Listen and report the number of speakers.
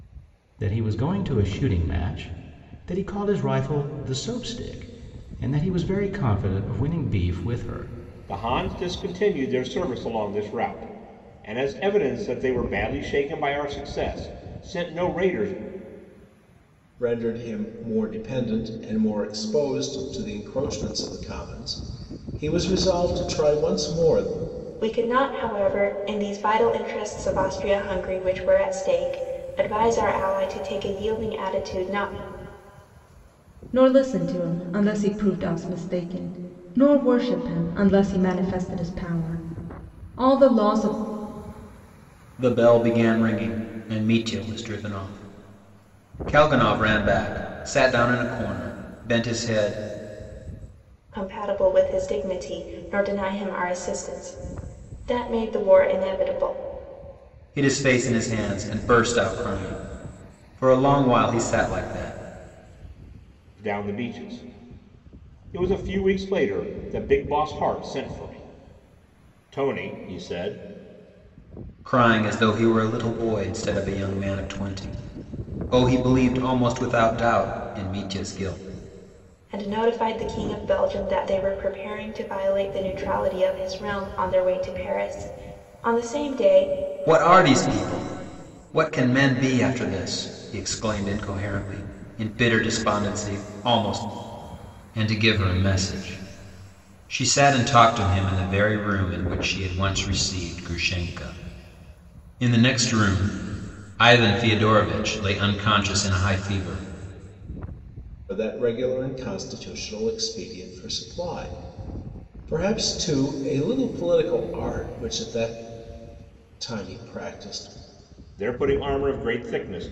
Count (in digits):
6